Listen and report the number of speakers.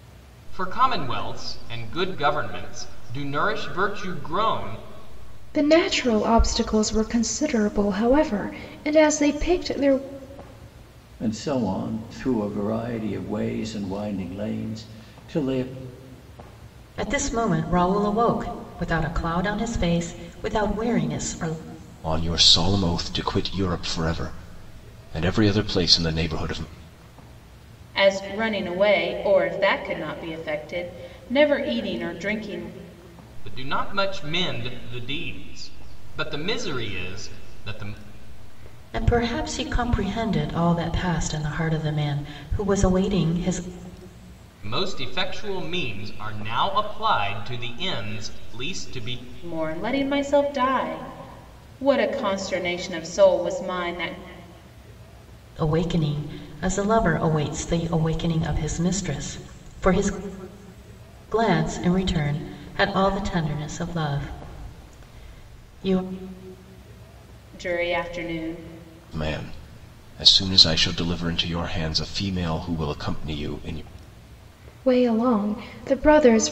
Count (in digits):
6